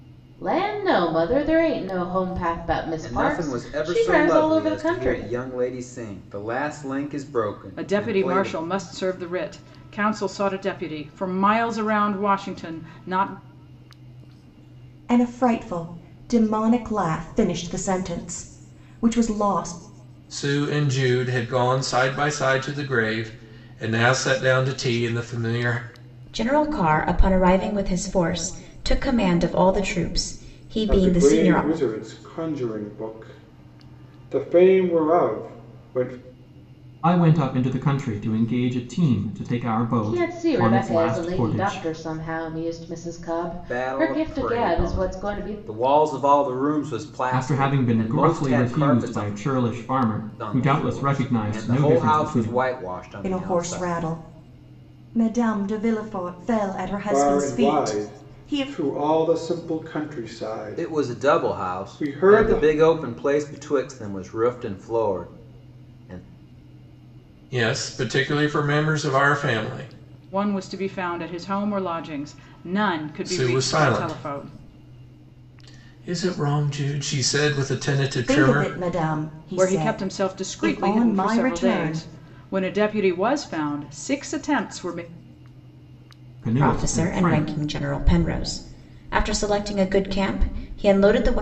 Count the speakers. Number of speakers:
8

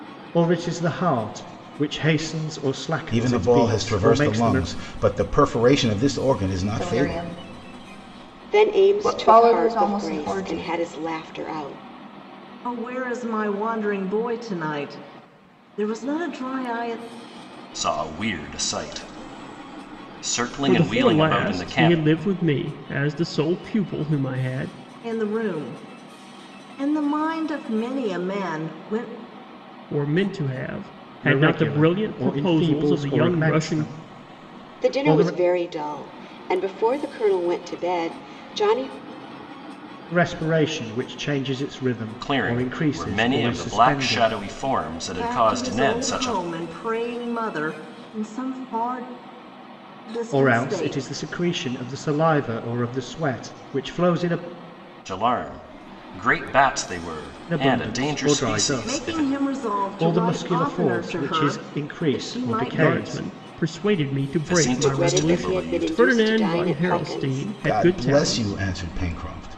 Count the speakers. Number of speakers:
7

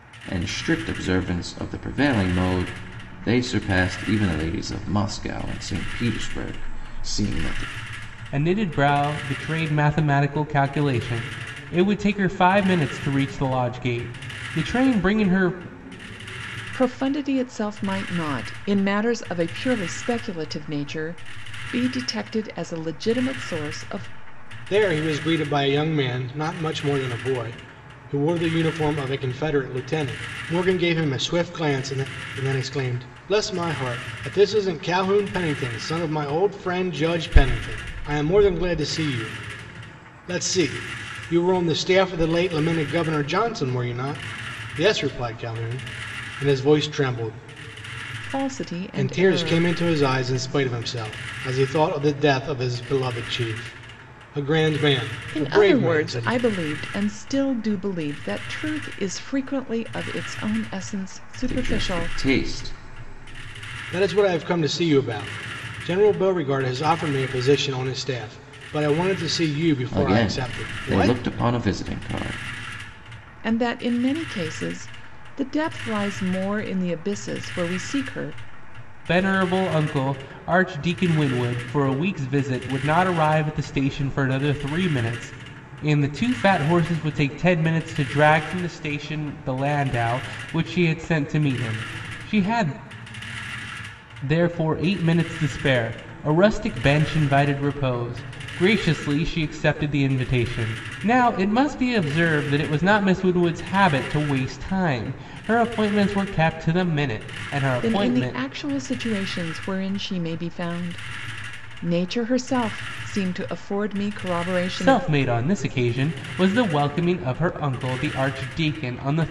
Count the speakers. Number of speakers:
4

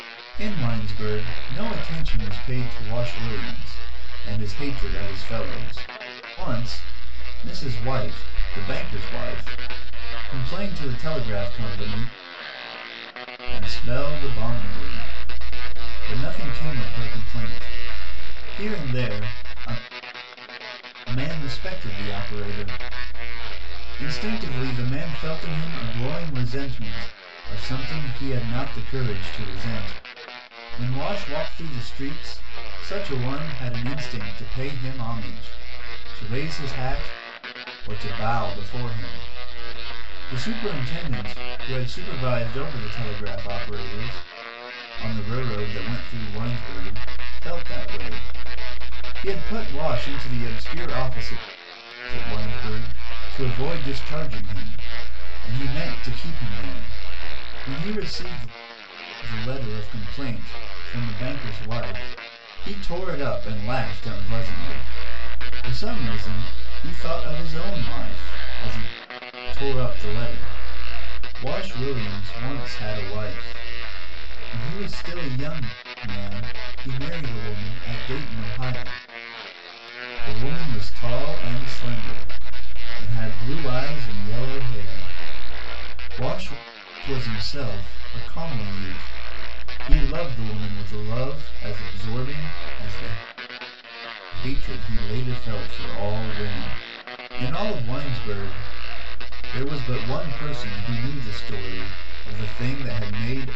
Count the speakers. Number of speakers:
1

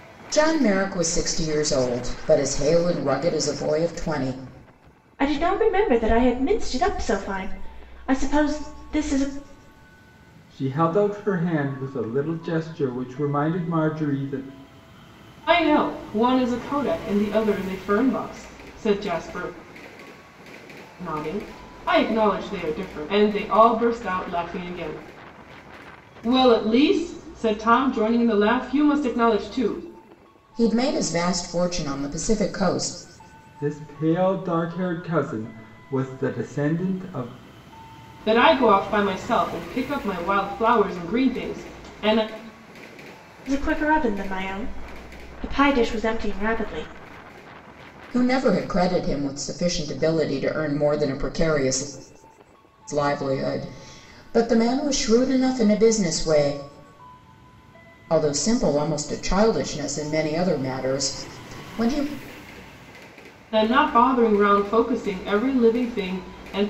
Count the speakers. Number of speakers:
4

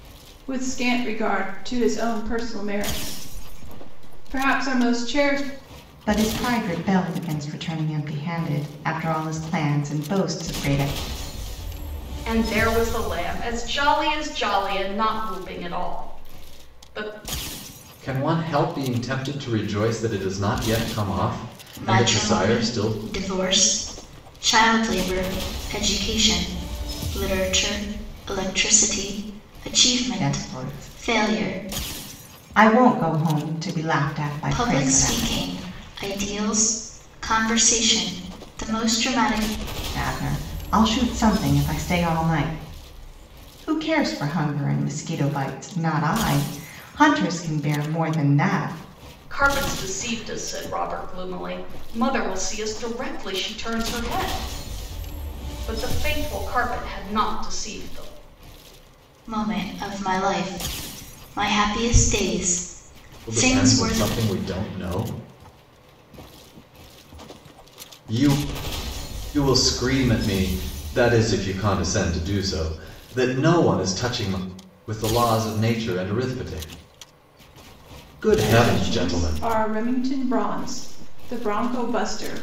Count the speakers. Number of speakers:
5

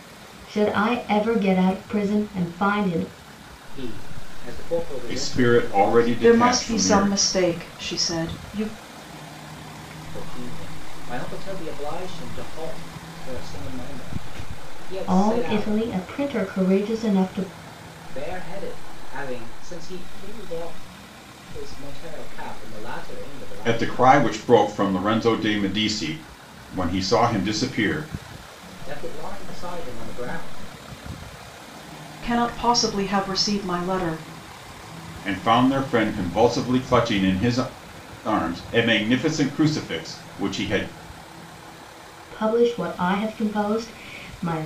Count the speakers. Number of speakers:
4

